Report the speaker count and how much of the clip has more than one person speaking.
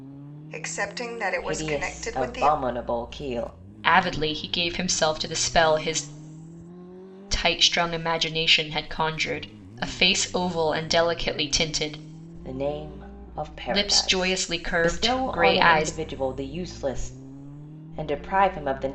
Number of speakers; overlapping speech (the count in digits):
3, about 16%